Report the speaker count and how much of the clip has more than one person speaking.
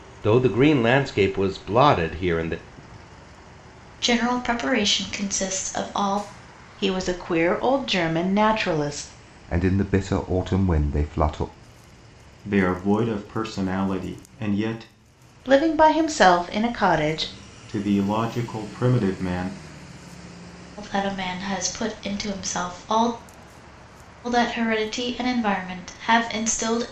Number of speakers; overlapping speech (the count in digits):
5, no overlap